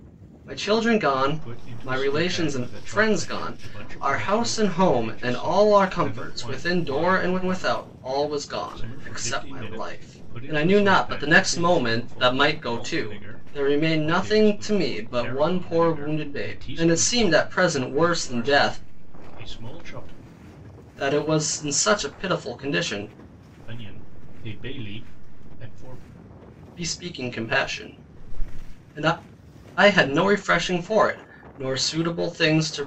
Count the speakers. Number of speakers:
2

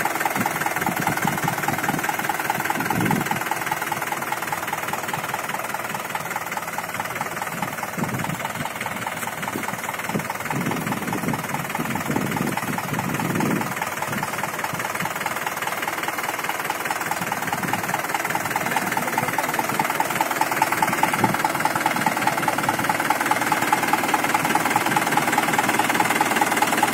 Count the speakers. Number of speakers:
0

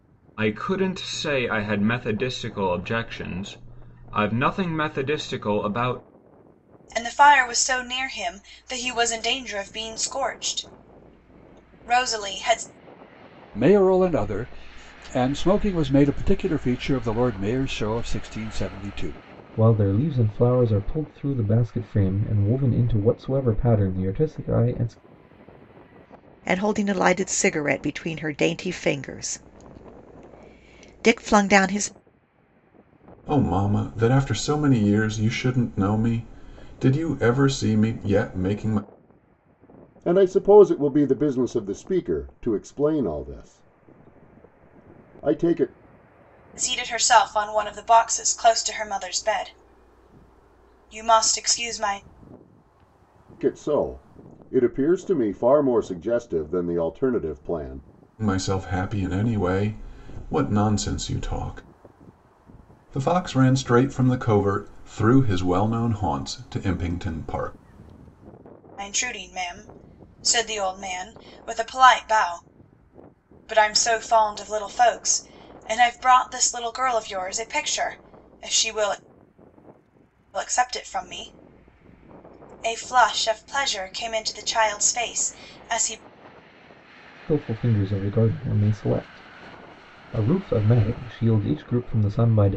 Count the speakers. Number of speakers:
7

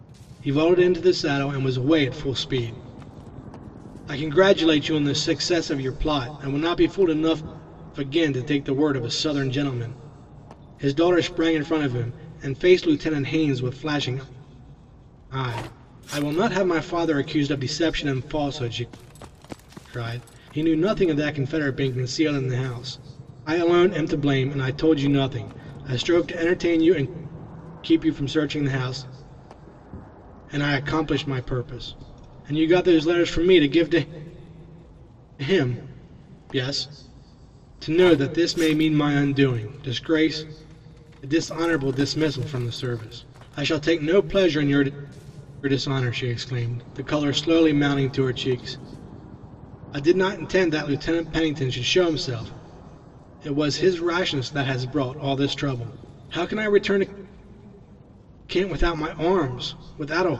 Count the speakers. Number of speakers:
1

